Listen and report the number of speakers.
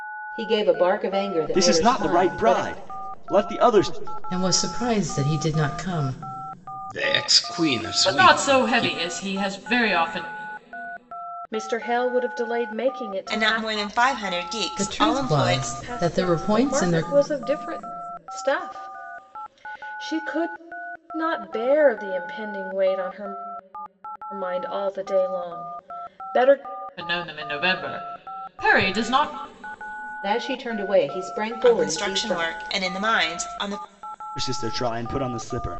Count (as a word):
seven